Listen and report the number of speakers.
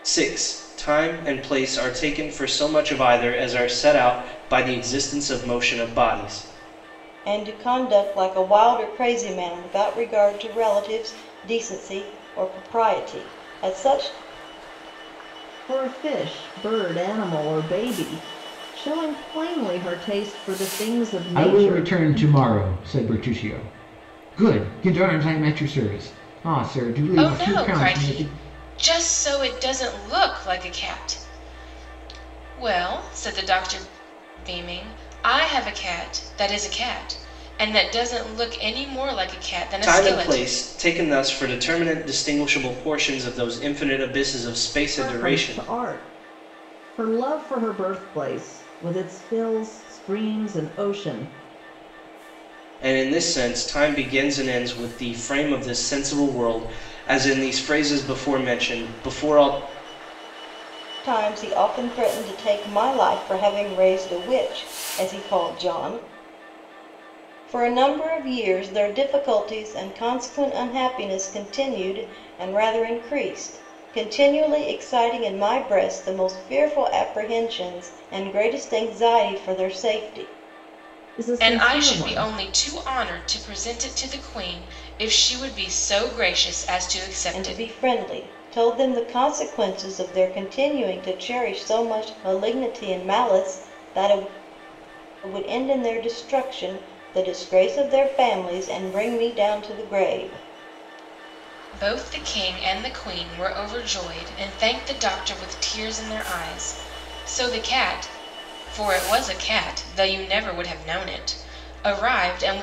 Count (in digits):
5